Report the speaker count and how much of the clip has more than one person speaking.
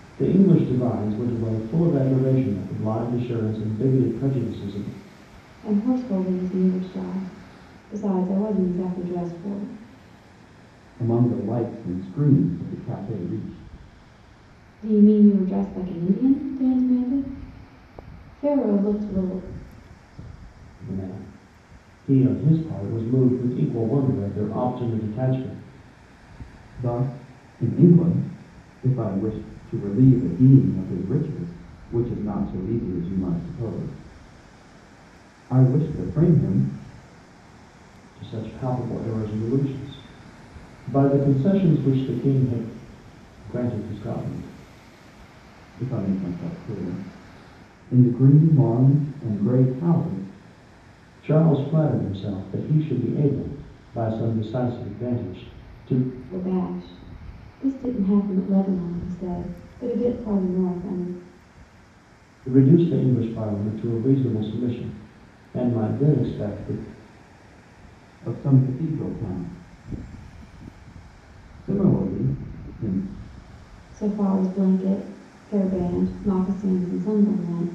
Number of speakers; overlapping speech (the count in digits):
3, no overlap